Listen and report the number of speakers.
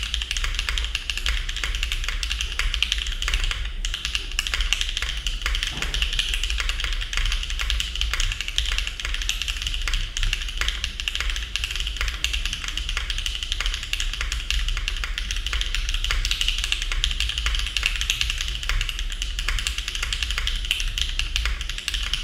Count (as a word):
zero